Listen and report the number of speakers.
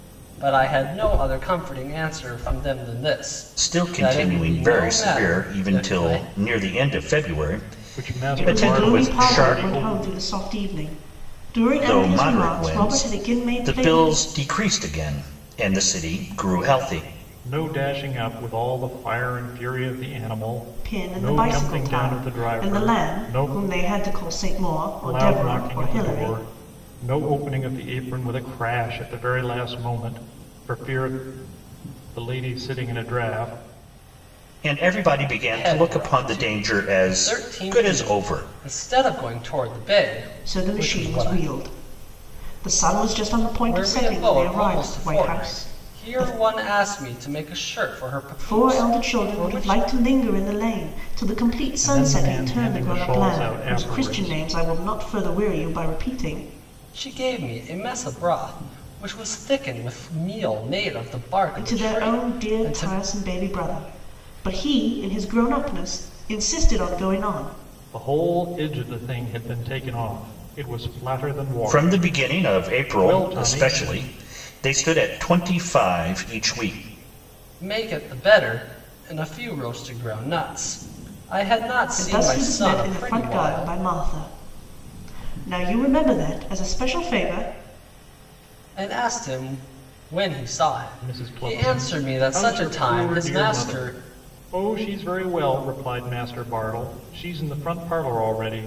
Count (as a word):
four